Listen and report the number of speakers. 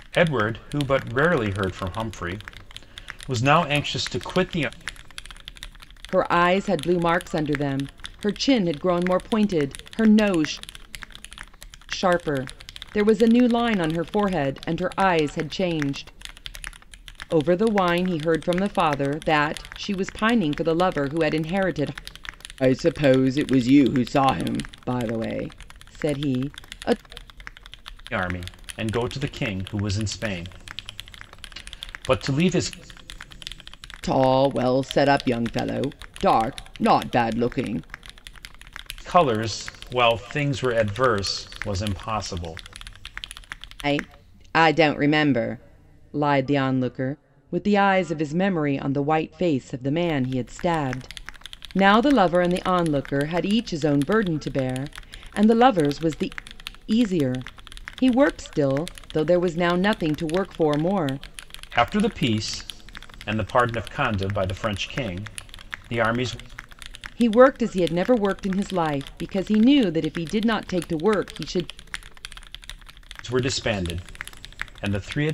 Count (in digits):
2